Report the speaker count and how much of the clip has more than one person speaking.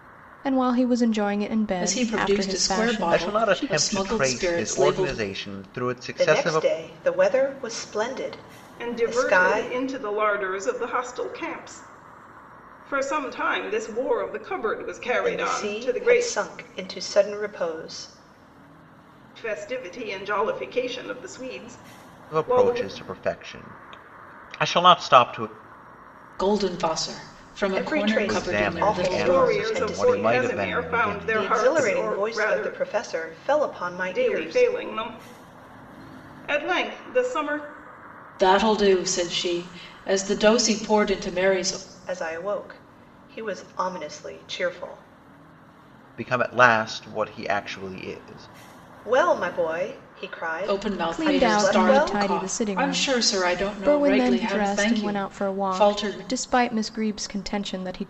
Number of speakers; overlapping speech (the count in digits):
5, about 31%